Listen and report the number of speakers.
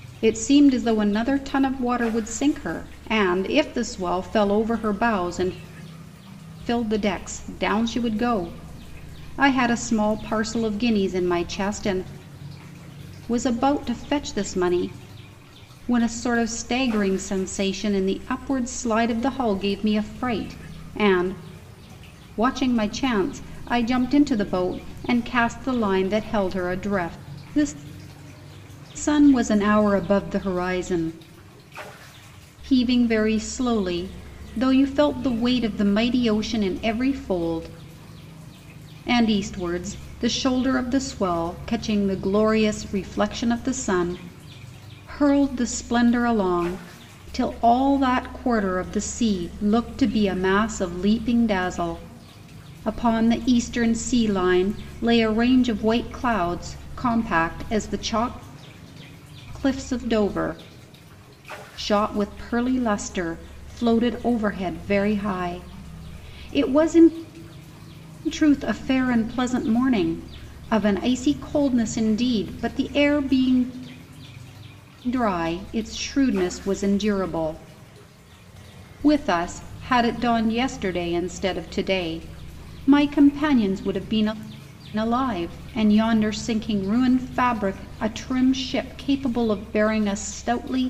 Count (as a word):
one